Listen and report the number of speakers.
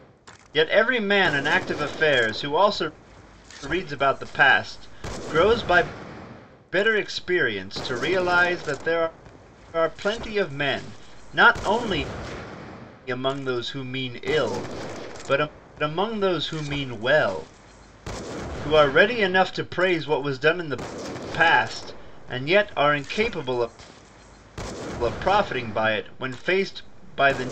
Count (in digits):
1